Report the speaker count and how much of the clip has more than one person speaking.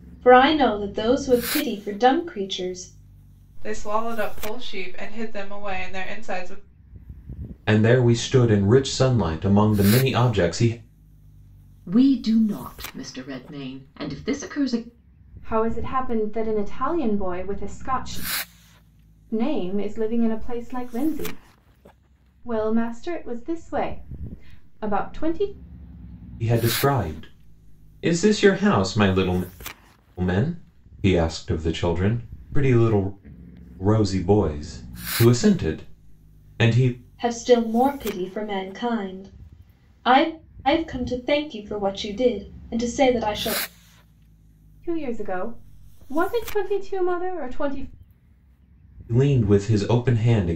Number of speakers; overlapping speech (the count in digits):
5, no overlap